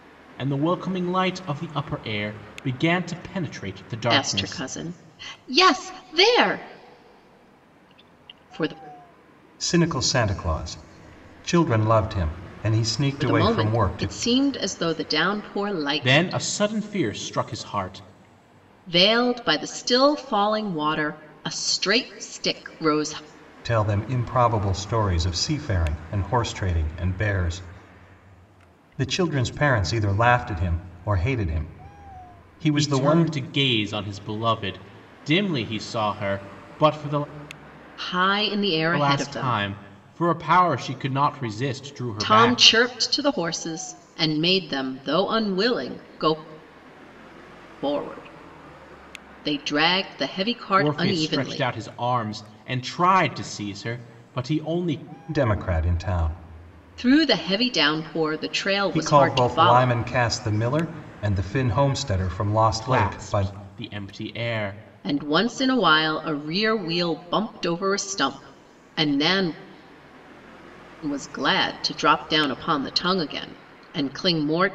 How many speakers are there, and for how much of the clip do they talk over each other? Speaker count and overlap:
three, about 9%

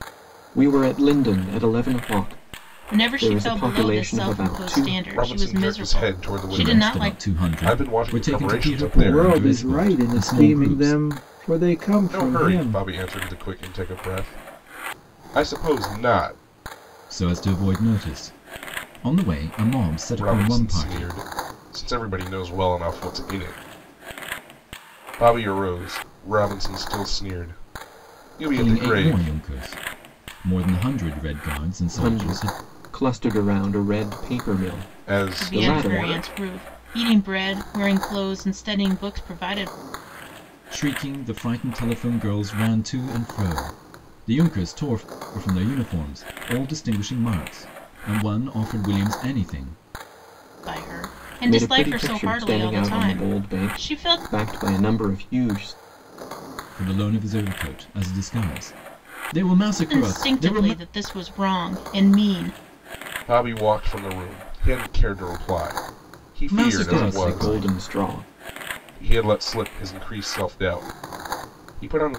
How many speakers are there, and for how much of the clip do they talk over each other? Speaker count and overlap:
five, about 24%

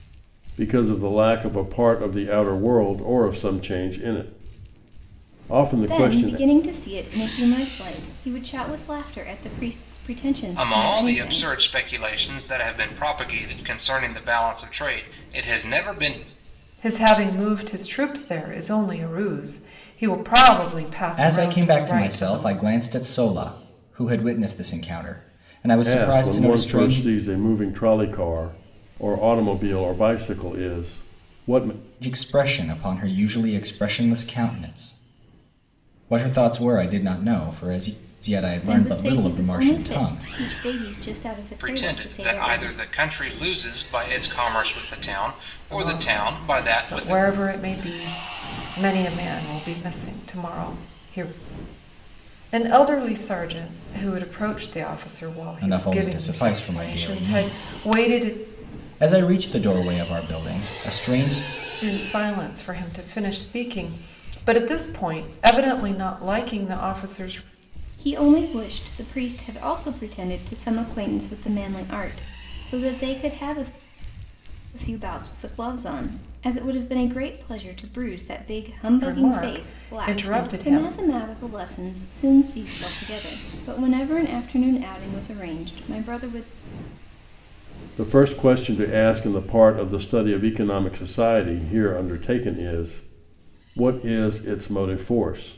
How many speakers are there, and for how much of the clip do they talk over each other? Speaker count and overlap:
five, about 14%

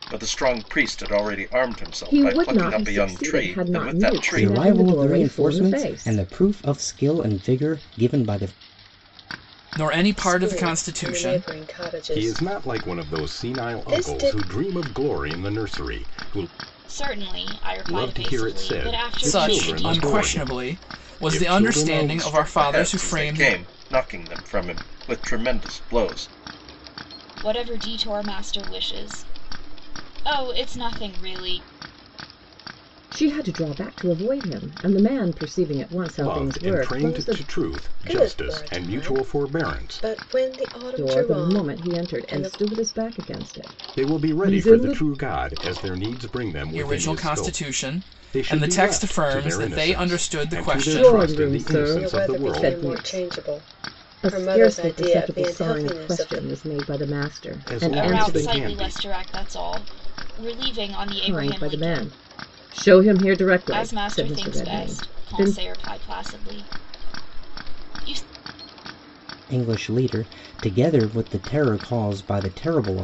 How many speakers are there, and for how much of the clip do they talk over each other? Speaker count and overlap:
seven, about 44%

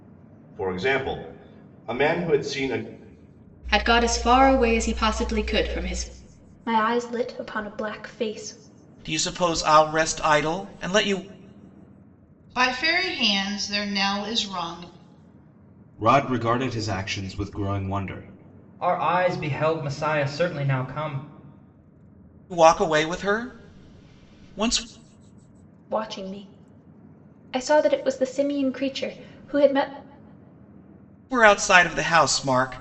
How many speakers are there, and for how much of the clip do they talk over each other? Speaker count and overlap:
seven, no overlap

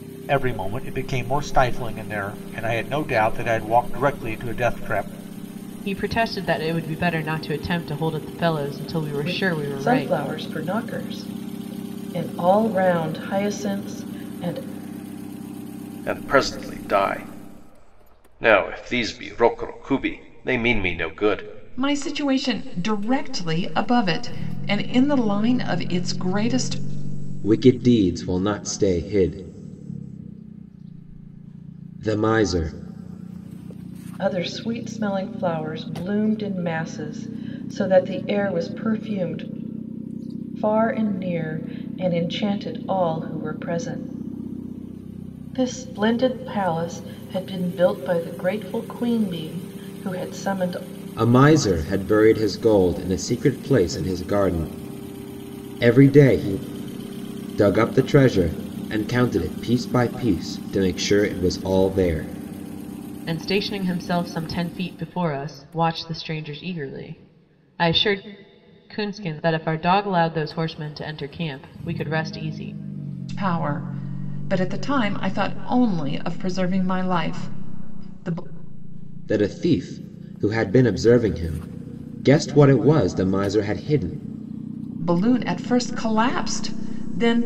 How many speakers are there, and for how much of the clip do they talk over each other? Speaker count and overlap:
six, about 1%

